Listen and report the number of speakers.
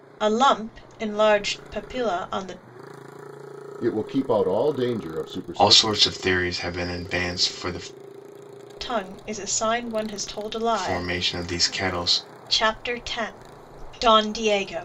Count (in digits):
3